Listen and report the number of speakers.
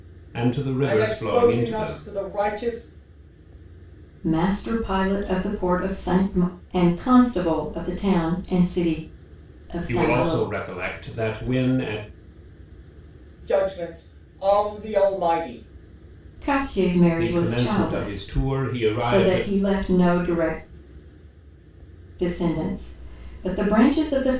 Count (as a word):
three